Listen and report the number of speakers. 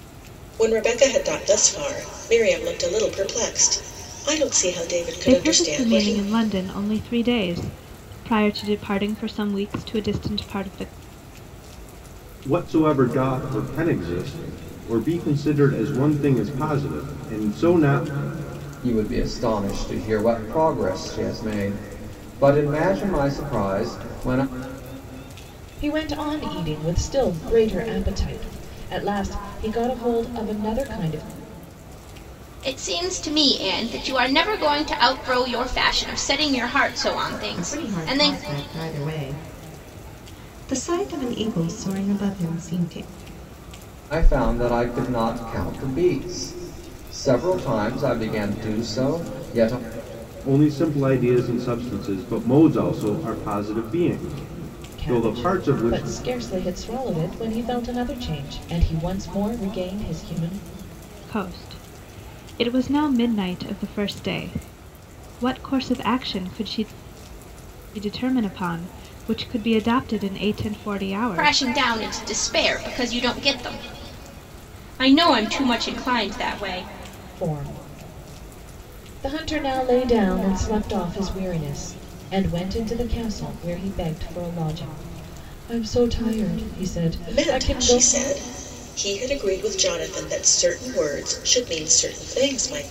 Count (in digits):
7